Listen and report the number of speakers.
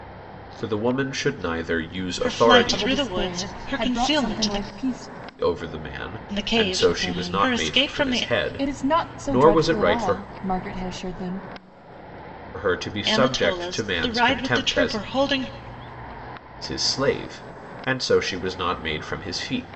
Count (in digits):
3